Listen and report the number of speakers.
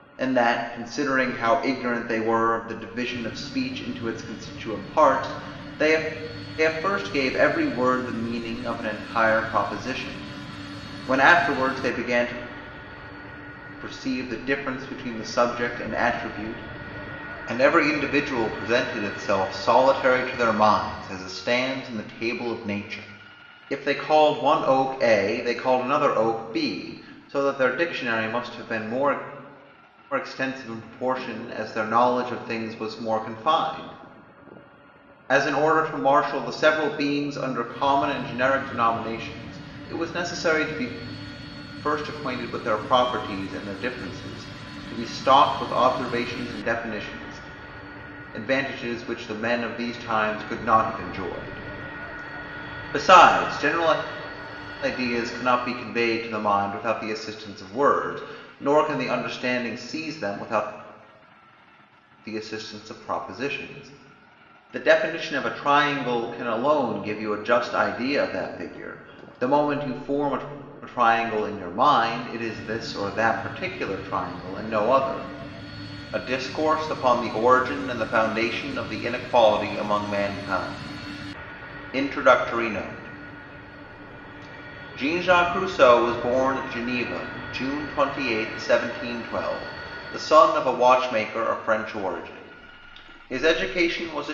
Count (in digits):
1